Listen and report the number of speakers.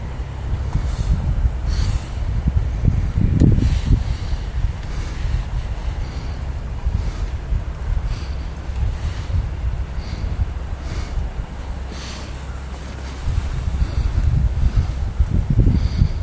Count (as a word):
zero